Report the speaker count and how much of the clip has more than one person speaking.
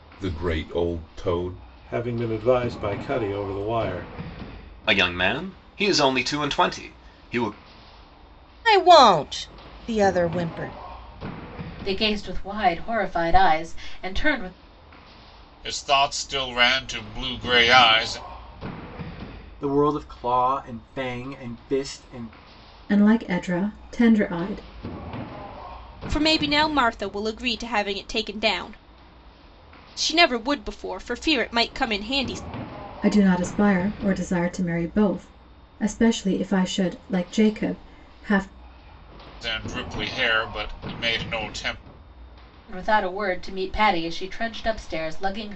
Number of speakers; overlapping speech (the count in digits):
9, no overlap